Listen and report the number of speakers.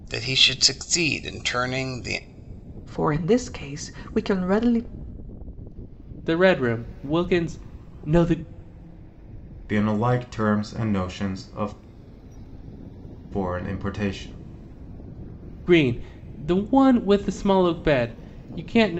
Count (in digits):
4